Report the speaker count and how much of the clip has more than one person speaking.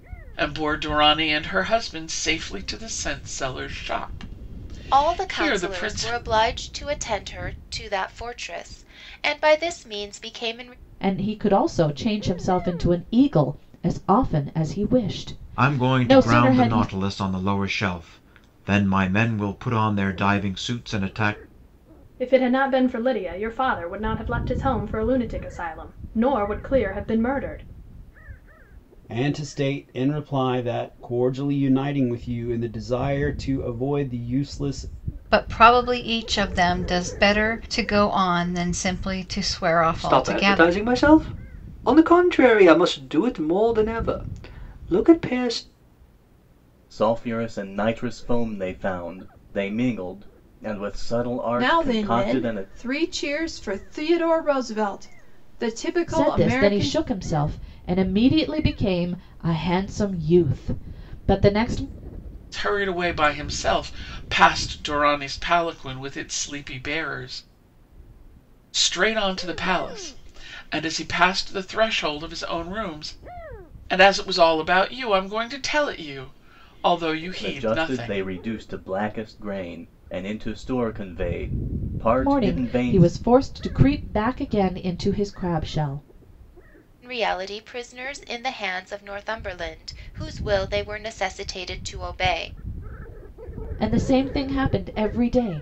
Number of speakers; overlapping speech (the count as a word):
ten, about 8%